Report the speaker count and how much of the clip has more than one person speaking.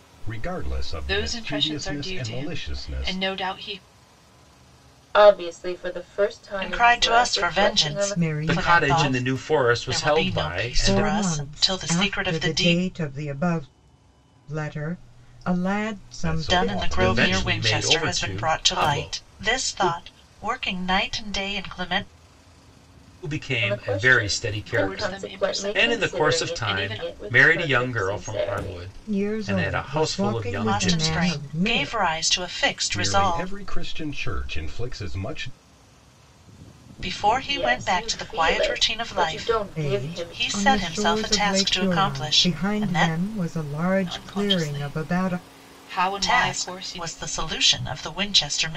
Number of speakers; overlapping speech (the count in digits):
6, about 58%